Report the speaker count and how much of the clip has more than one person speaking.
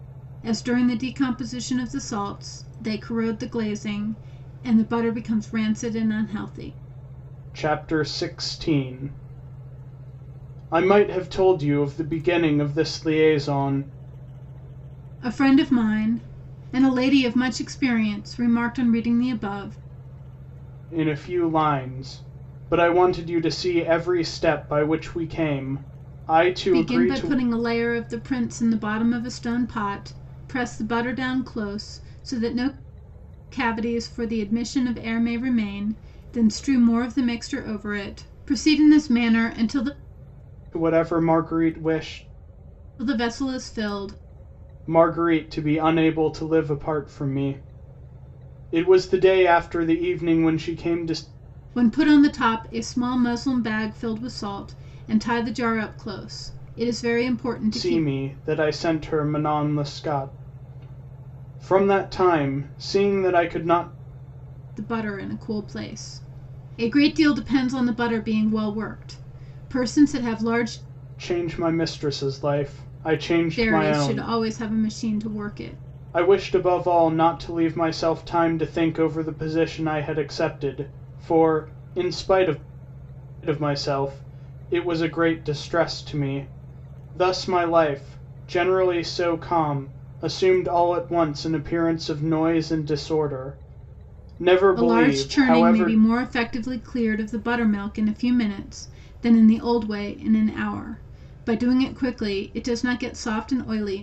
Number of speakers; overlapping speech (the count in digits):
2, about 3%